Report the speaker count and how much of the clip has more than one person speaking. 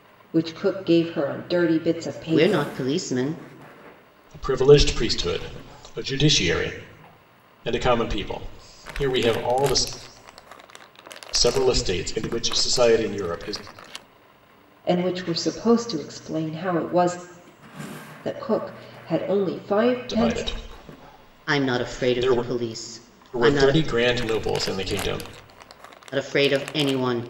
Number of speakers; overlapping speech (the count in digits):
3, about 9%